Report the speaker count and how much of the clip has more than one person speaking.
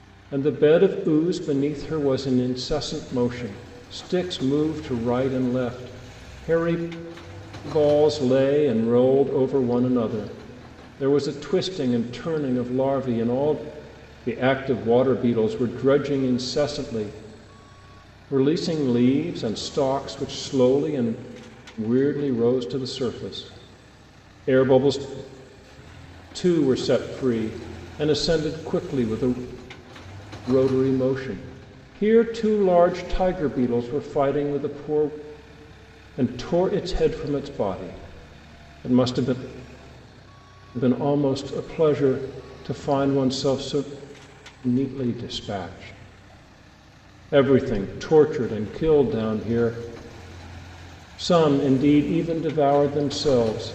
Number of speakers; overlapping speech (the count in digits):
1, no overlap